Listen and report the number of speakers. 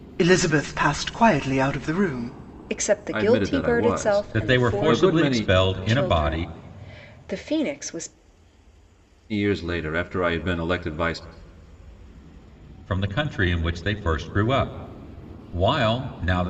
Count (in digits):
4